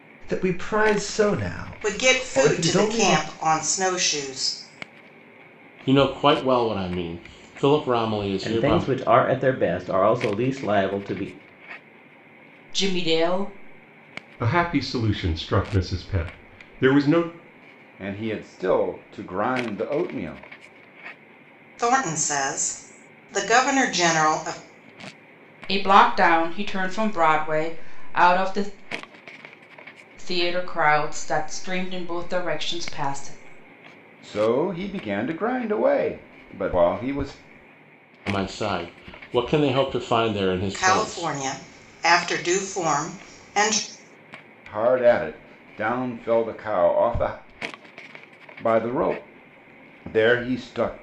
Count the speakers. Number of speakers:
seven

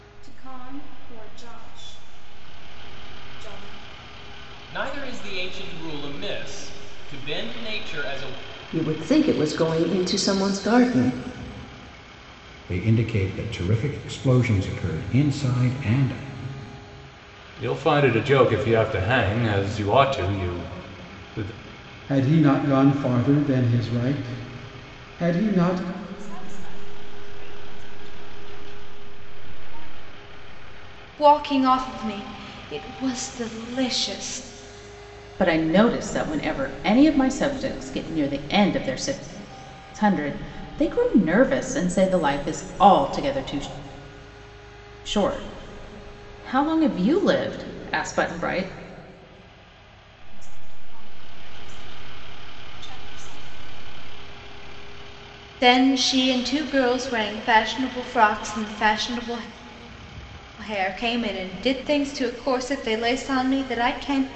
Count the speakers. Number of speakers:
nine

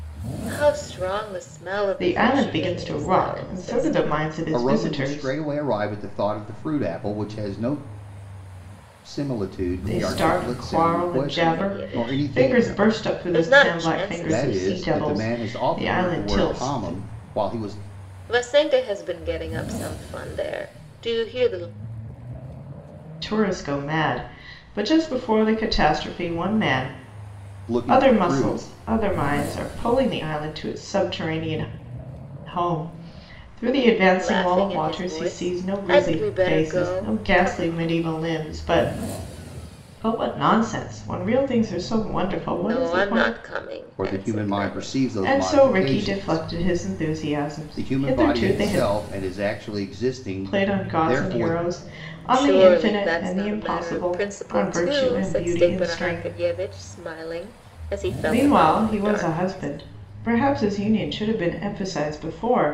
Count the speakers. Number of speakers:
three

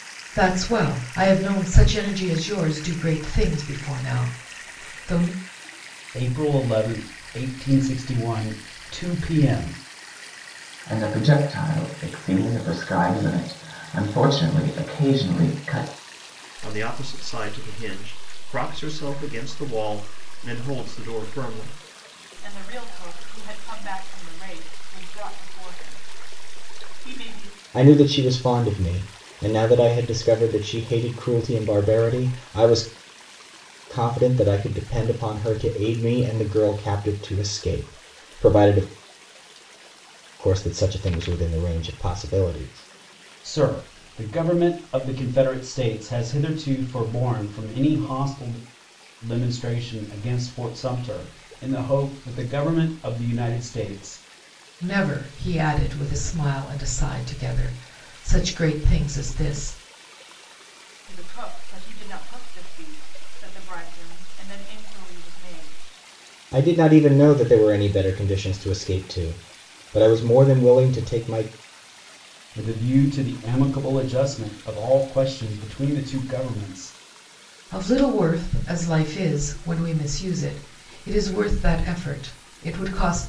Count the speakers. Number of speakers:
six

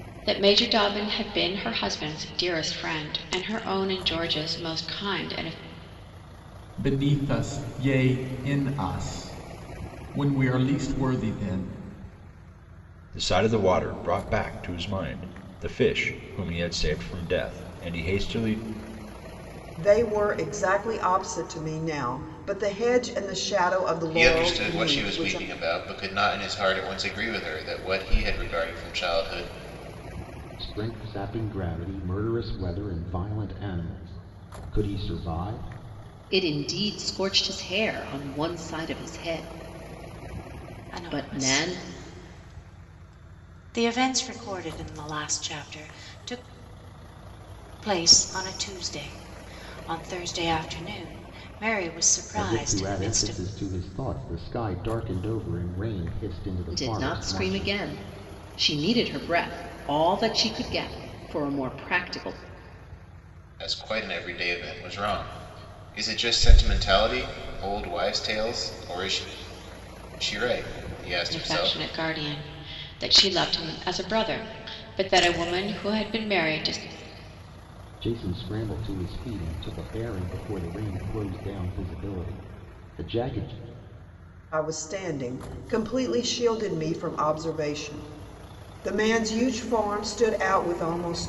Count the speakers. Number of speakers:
eight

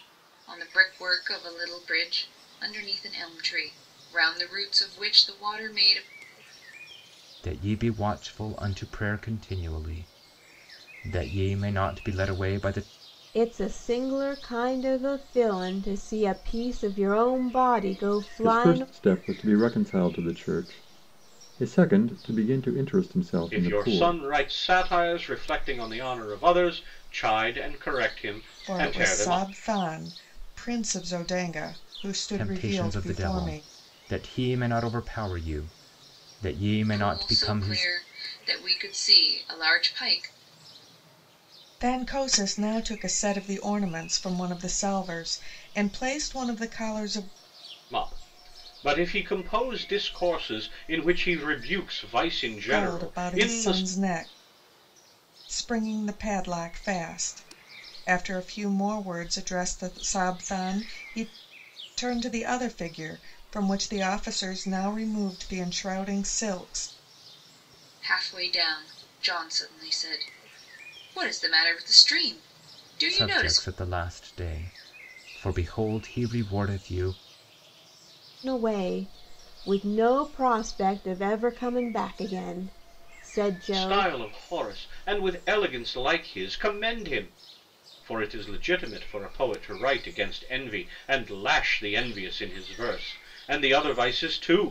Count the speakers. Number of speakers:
six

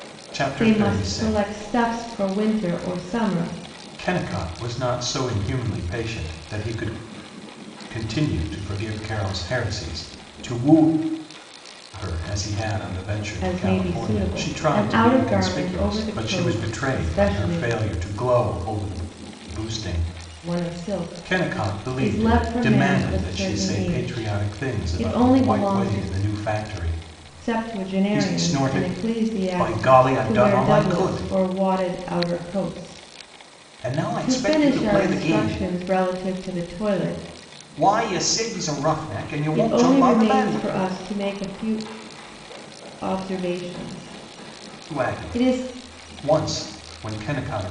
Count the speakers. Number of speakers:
two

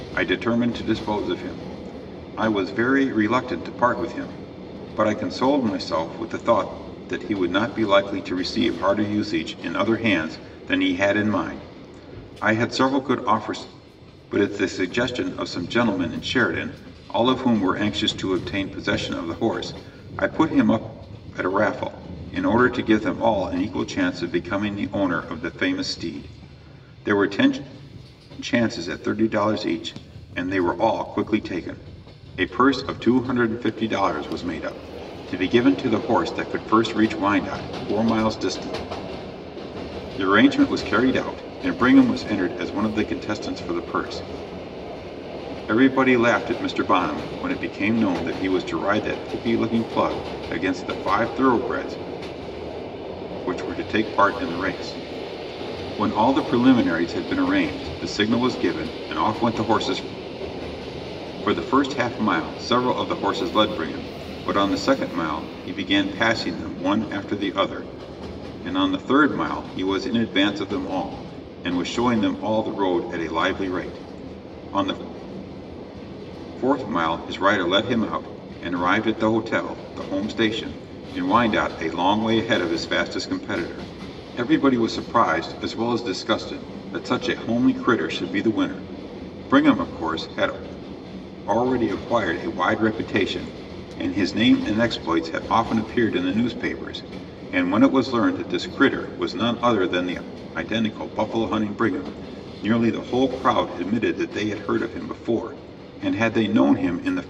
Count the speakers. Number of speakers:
one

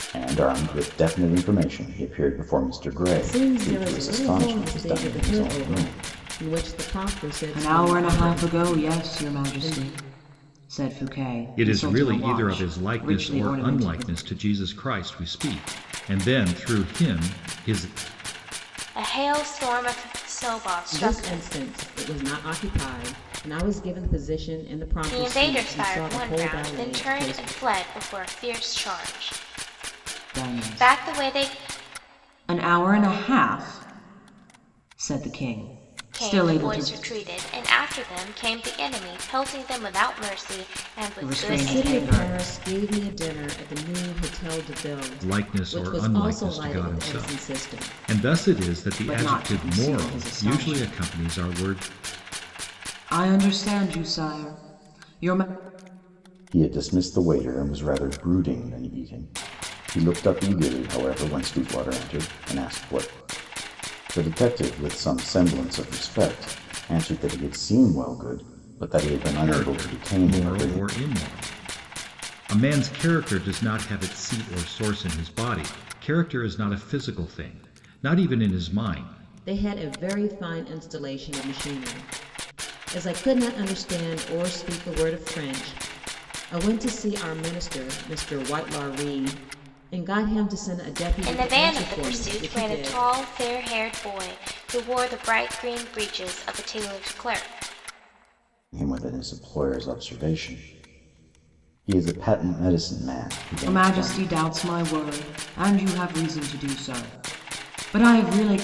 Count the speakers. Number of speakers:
five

